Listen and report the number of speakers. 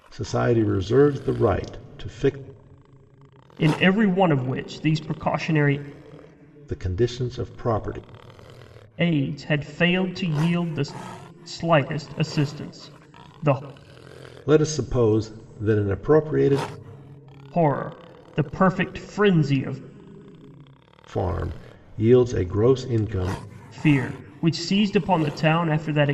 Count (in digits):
2